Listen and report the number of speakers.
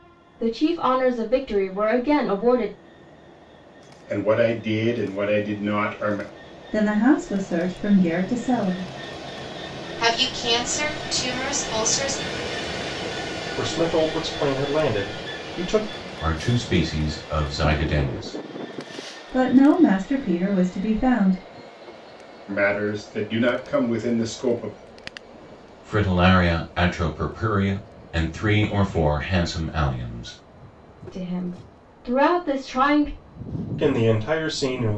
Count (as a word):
six